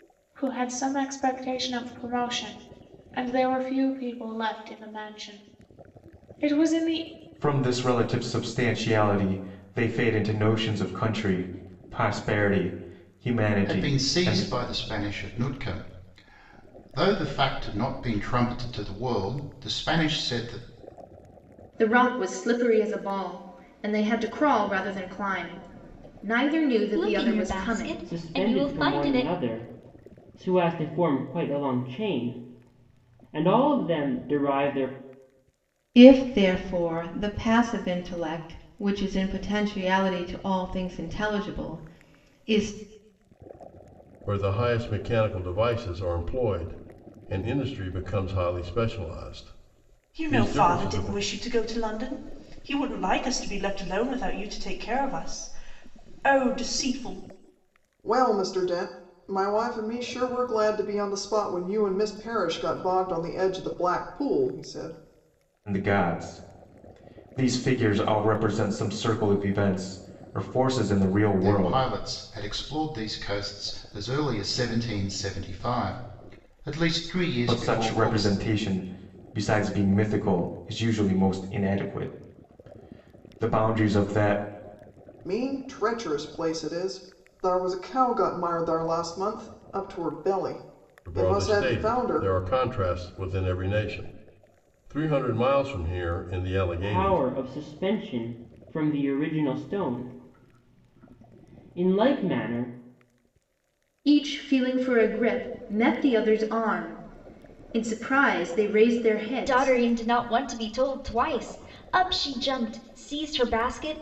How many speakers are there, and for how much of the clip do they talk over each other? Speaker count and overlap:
10, about 7%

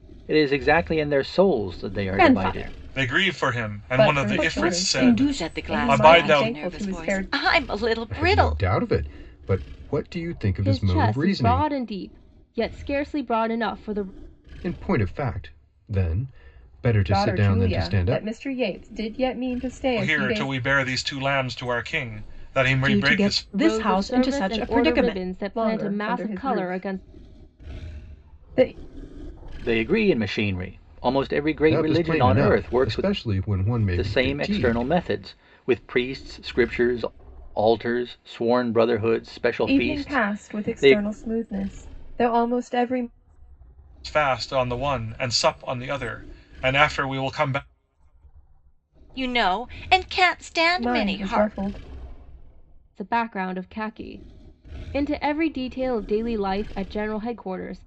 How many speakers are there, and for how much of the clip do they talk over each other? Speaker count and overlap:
7, about 30%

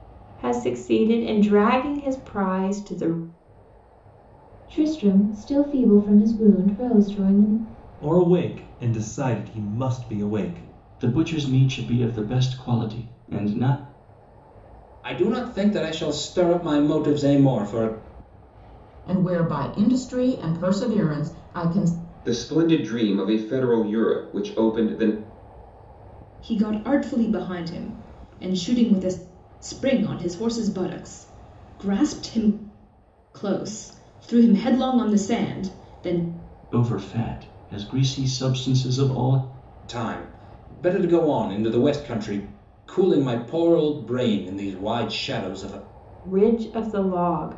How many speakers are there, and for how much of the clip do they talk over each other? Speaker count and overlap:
8, no overlap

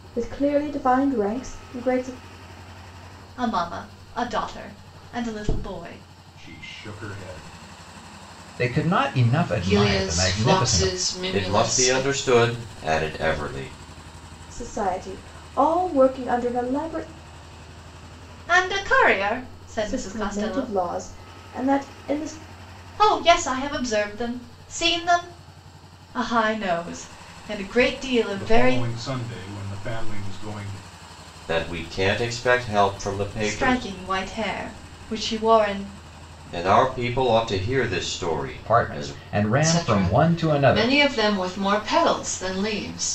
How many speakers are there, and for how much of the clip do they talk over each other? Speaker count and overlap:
6, about 14%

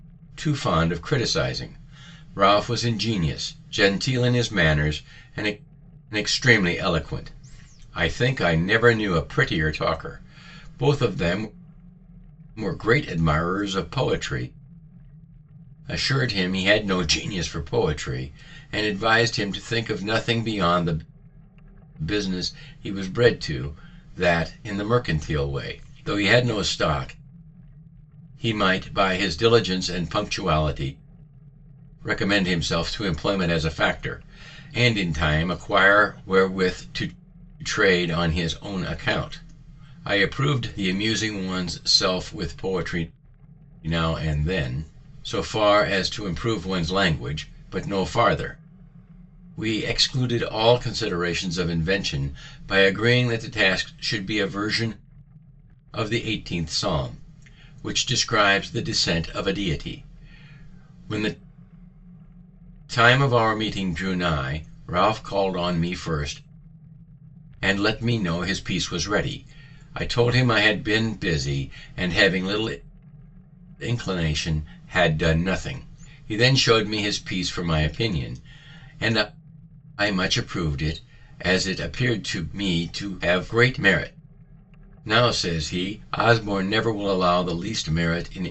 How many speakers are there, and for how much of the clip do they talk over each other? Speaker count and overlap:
1, no overlap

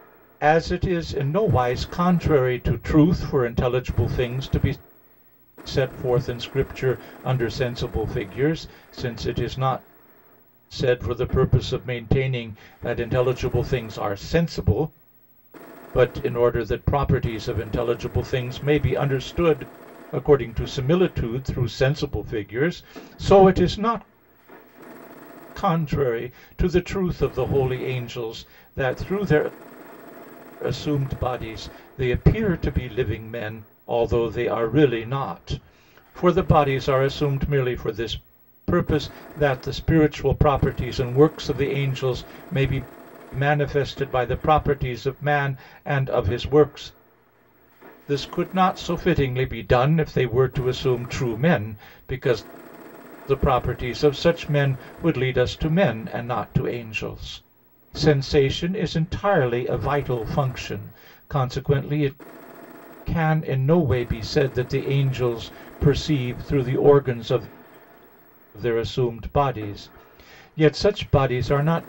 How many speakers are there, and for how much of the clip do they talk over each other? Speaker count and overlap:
1, no overlap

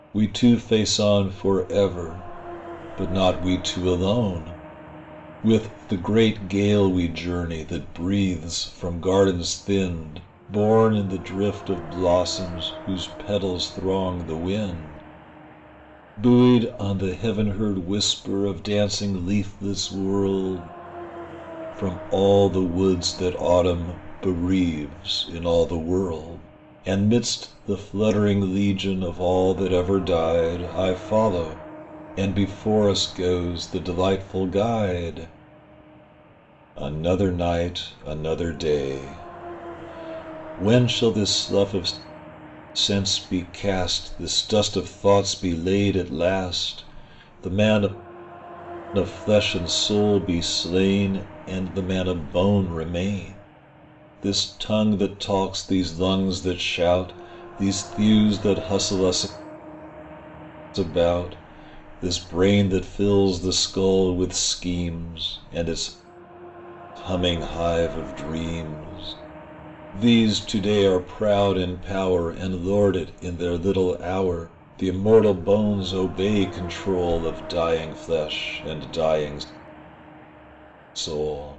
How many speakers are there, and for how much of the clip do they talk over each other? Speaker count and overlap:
1, no overlap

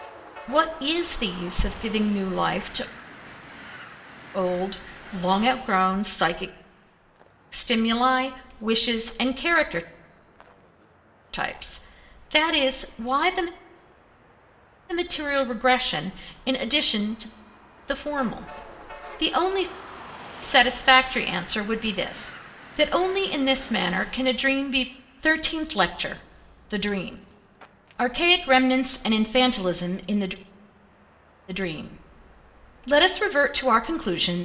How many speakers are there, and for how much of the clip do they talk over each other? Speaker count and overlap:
1, no overlap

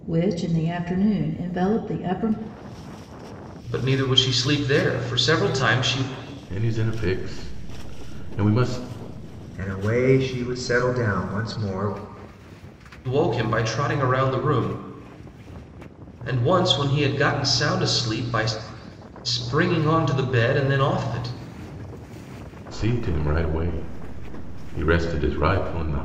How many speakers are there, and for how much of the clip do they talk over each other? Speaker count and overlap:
4, no overlap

